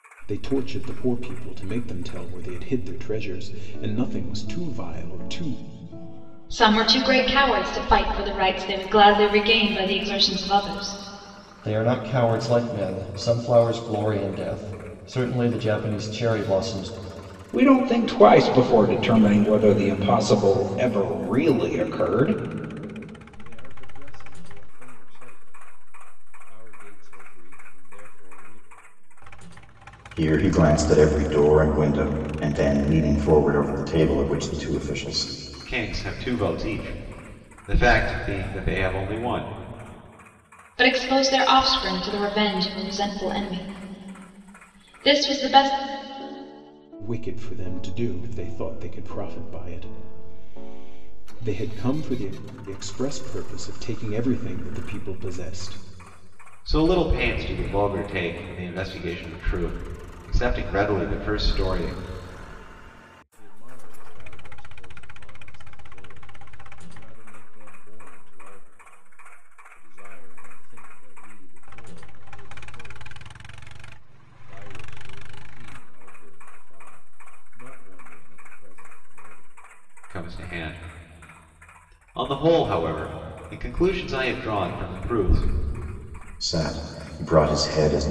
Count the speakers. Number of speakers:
7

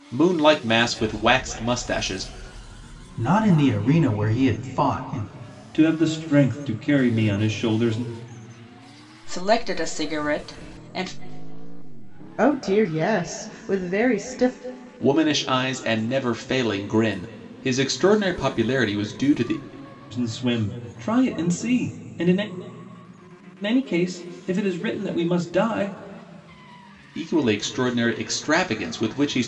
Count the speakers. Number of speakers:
5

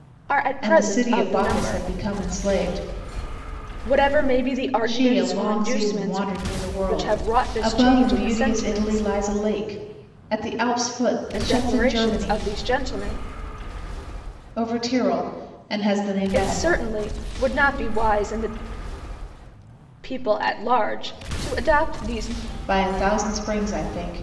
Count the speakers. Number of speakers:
2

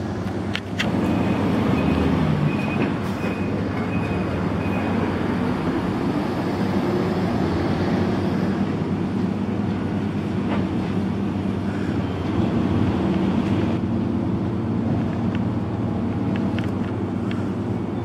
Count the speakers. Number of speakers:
0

